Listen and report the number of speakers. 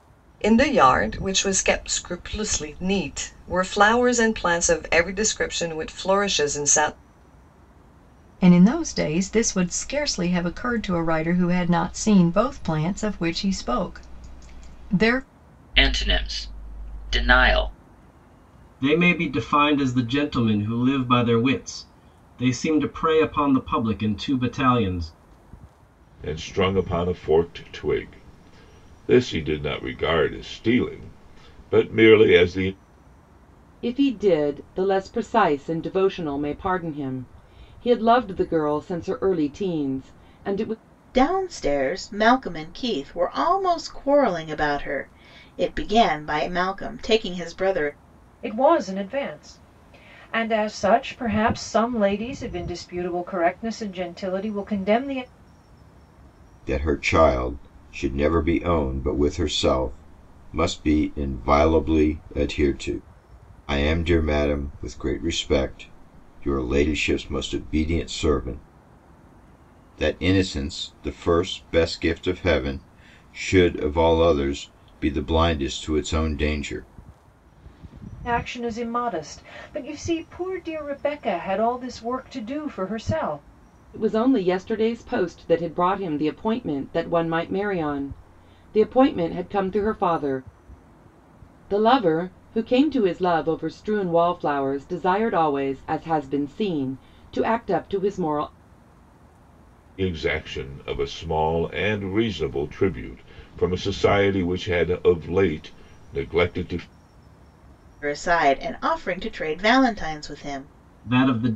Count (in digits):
9